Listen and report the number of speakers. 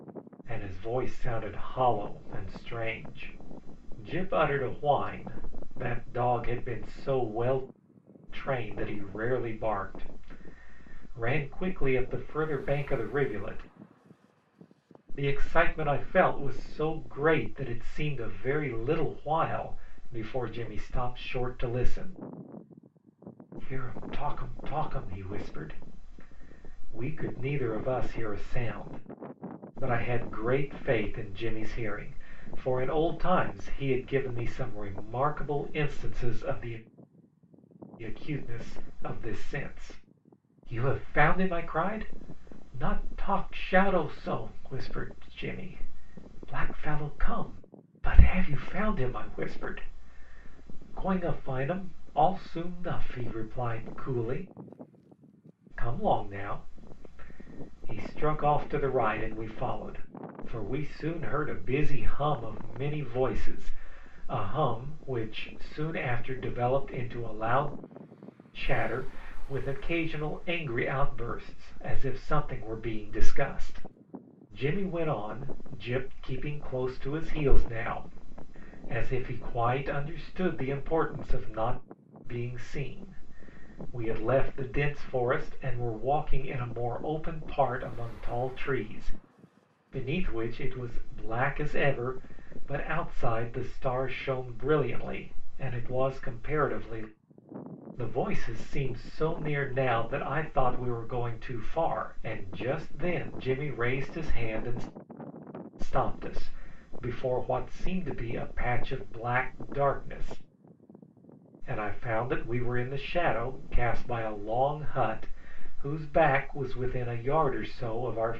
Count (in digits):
1